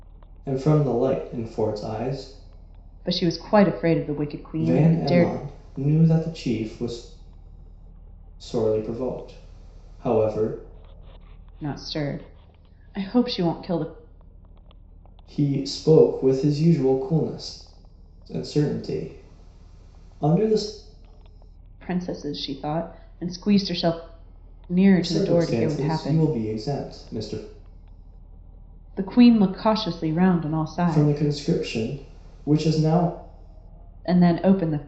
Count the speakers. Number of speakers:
two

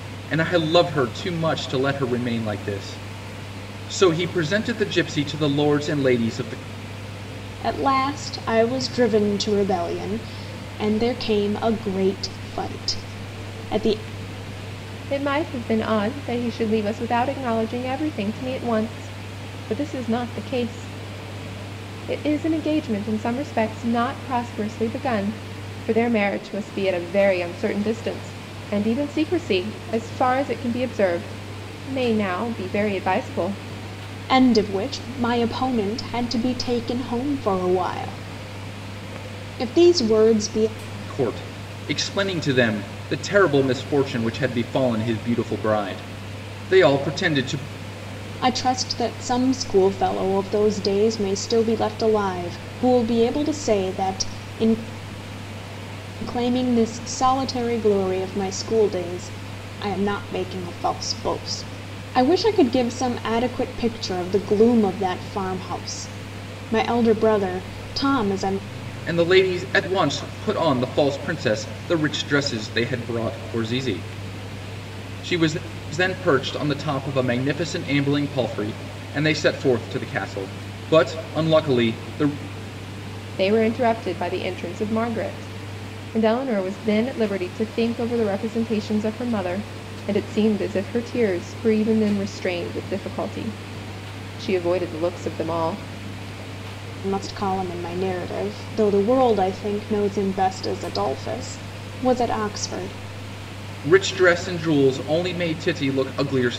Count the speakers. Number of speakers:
three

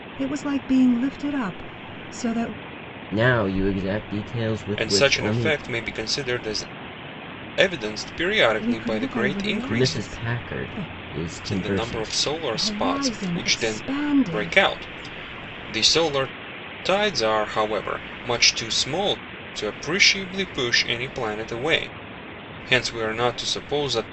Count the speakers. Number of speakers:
three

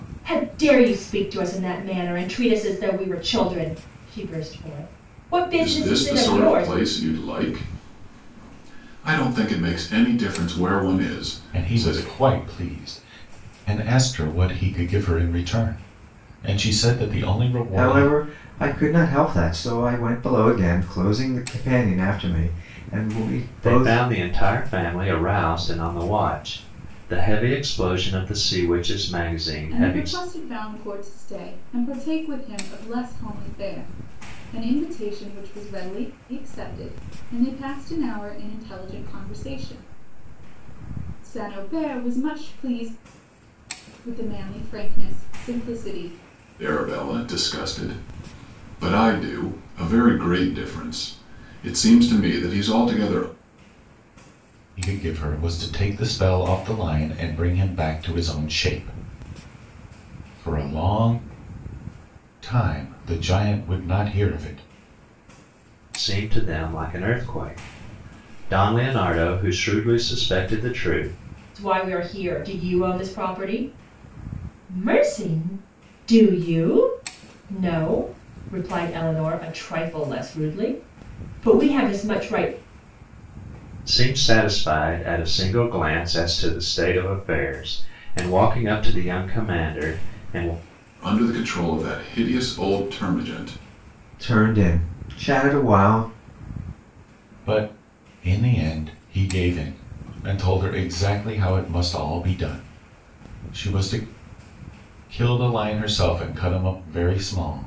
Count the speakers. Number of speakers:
six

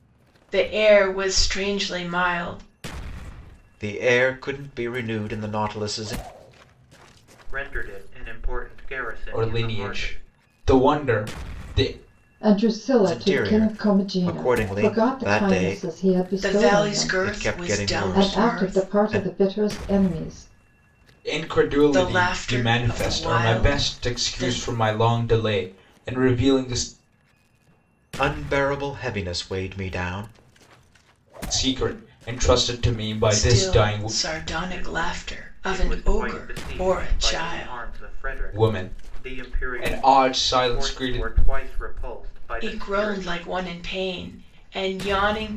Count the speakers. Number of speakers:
five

